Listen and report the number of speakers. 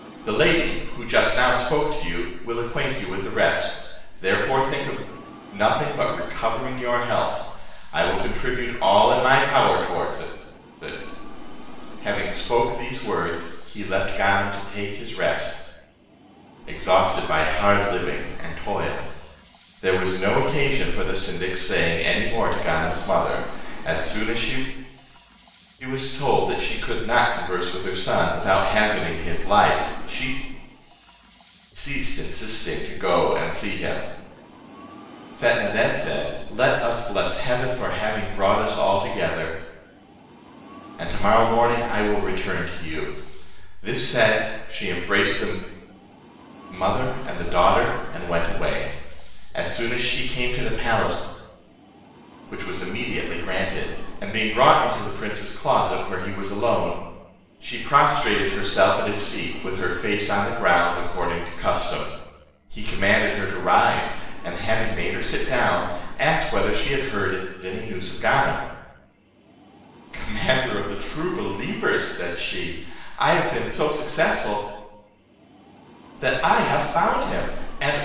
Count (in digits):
1